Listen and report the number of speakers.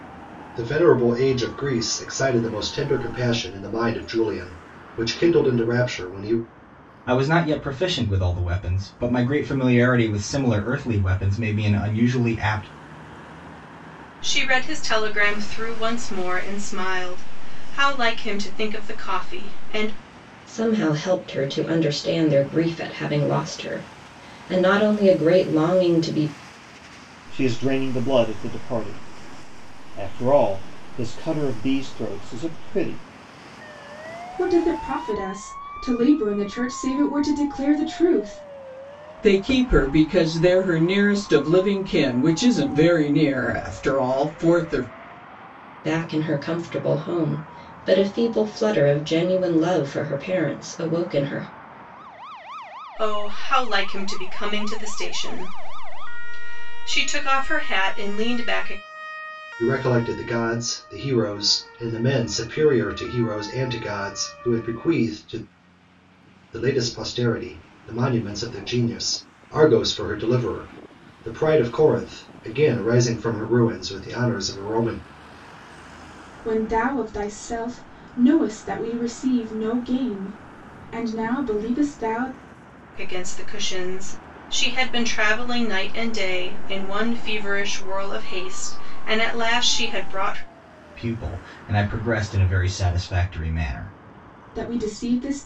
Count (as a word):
seven